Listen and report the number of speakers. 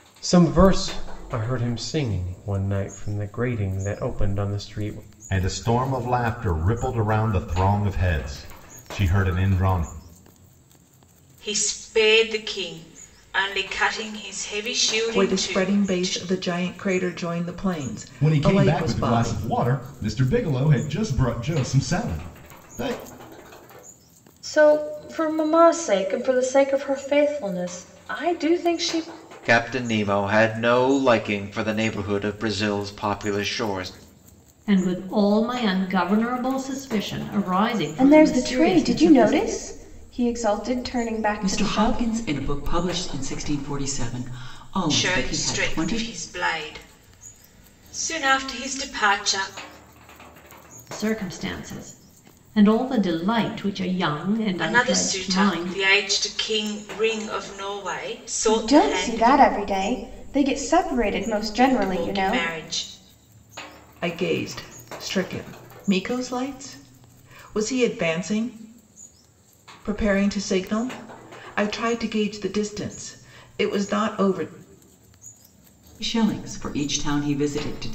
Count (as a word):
ten